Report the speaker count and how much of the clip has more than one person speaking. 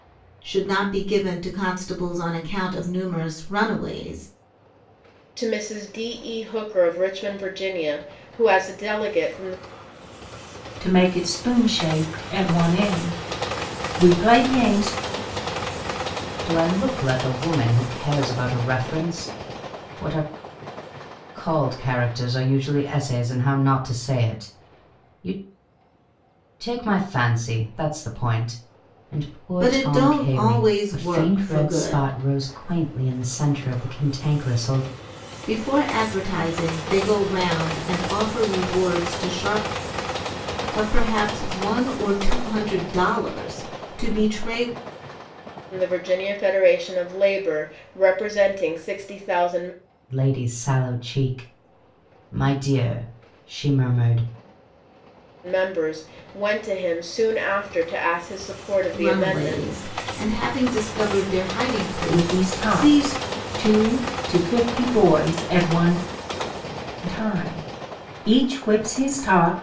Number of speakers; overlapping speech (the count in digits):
4, about 6%